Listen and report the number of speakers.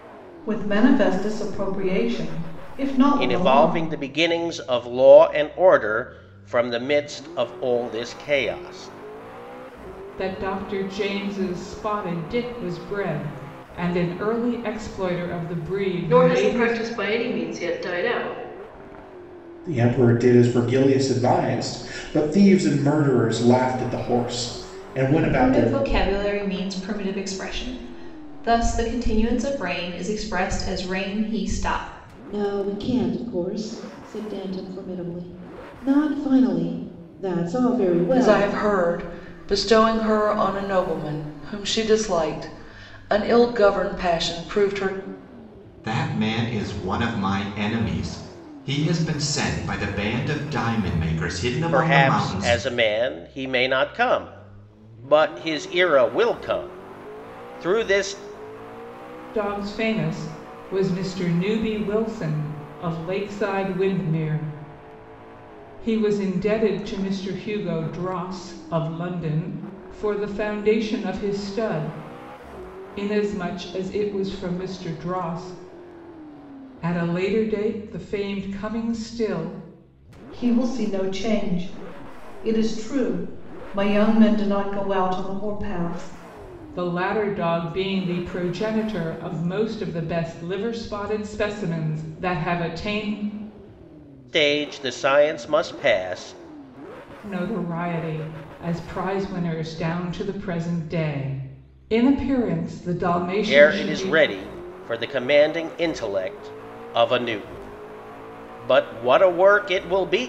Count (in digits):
9